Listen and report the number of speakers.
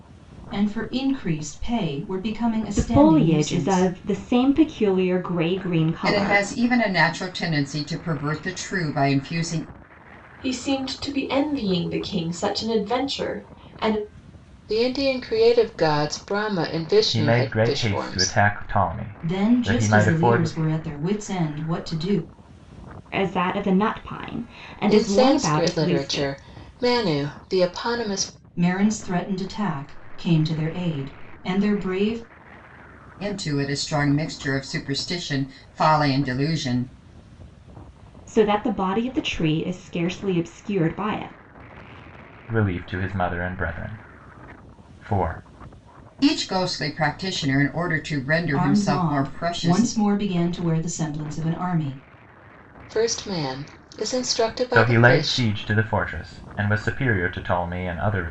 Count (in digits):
6